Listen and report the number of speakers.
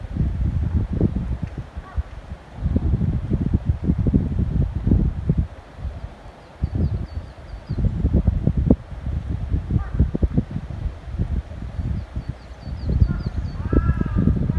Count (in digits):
0